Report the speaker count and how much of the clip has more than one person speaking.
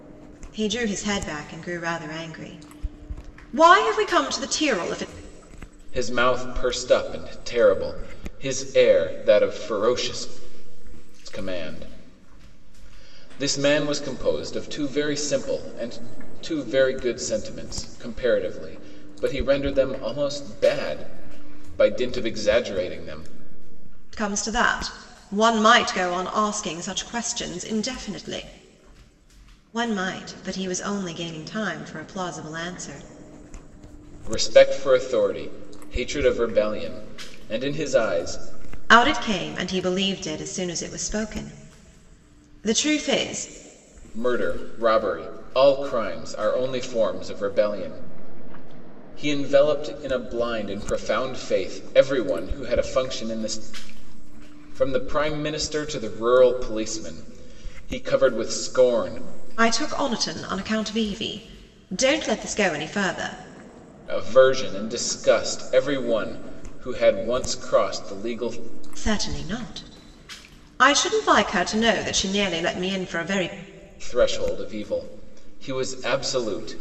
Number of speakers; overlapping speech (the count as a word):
two, no overlap